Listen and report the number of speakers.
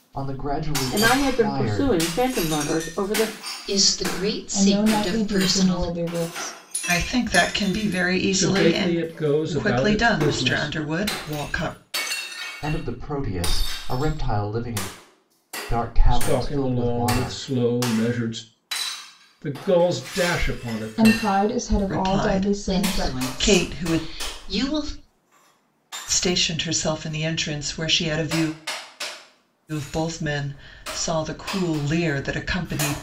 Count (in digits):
6